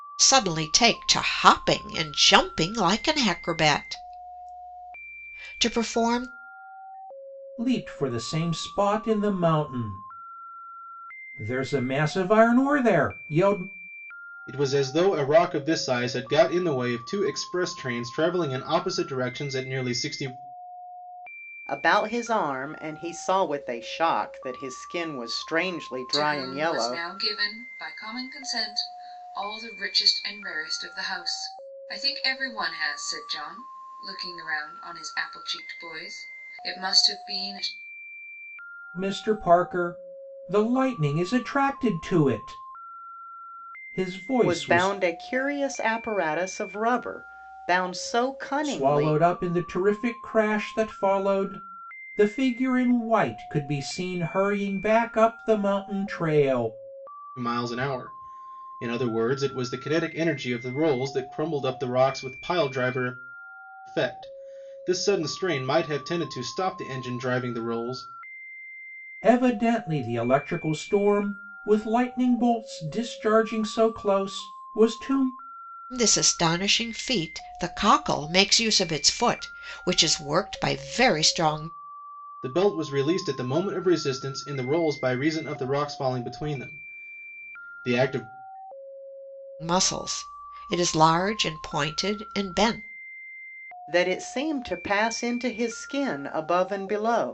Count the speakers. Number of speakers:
5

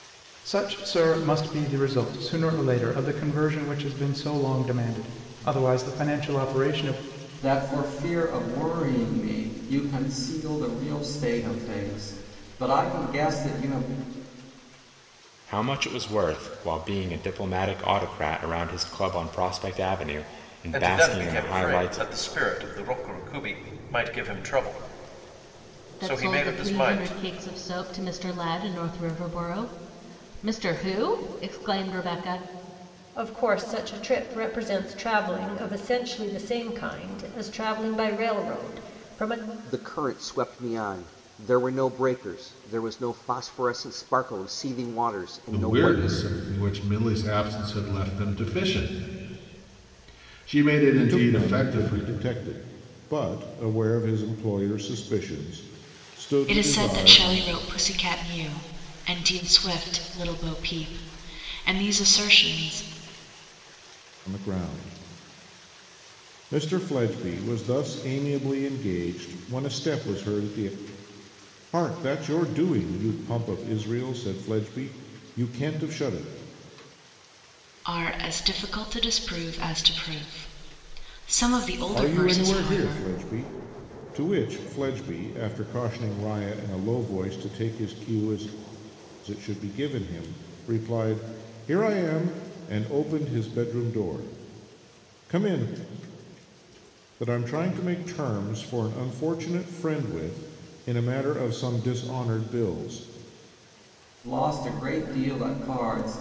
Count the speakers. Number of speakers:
10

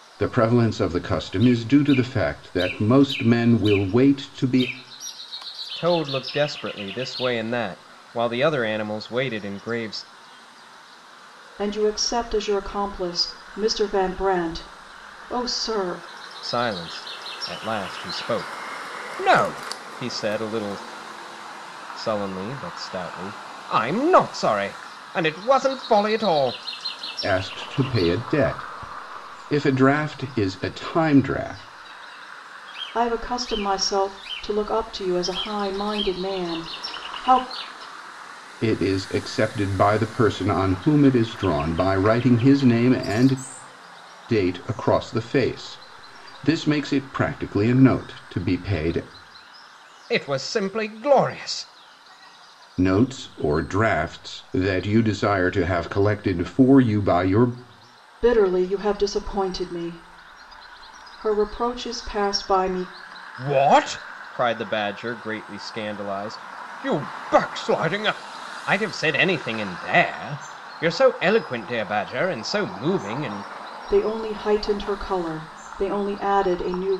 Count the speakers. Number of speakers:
3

